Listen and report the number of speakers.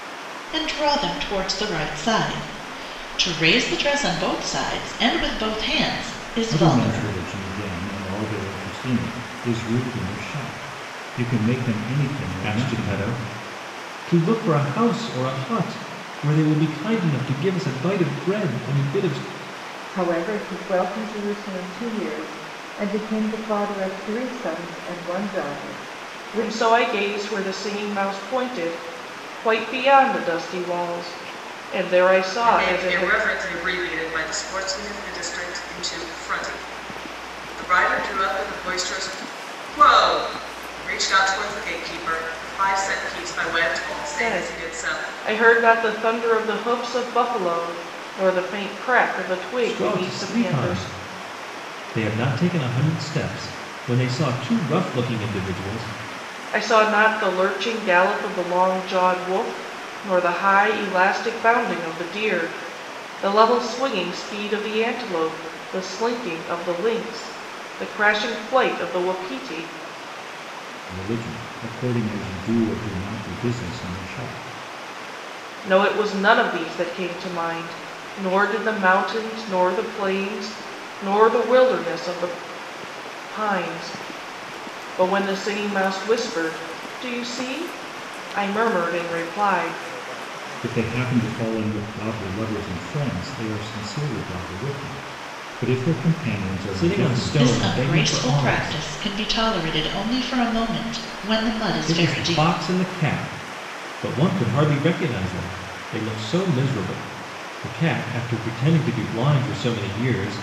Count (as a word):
six